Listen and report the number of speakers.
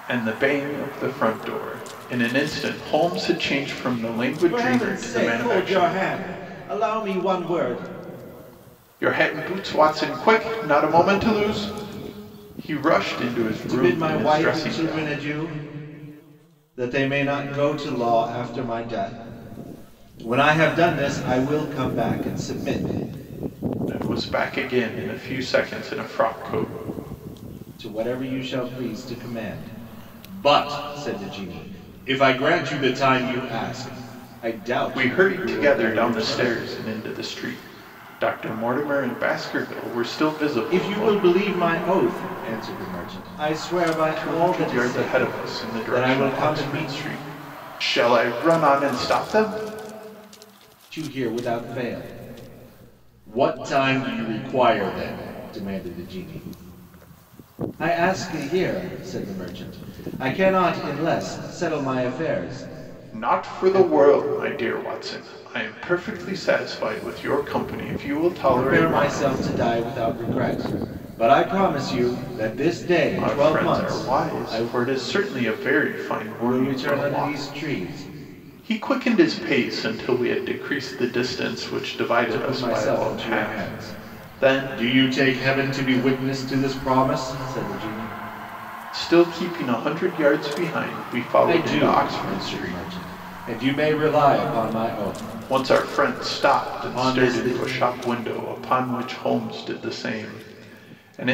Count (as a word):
two